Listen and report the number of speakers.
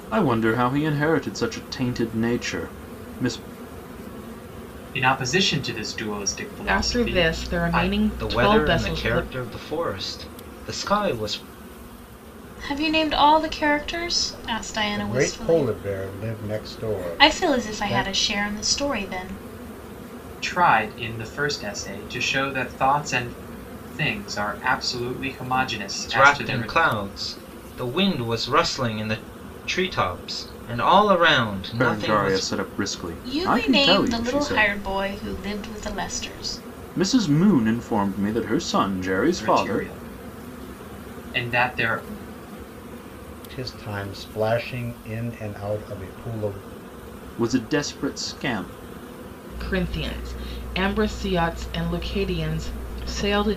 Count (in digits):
6